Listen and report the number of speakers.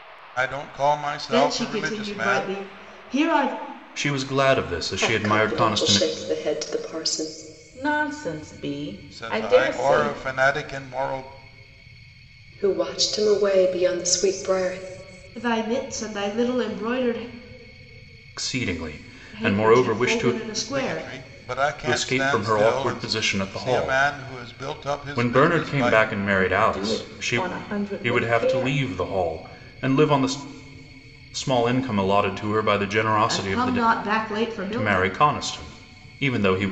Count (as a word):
five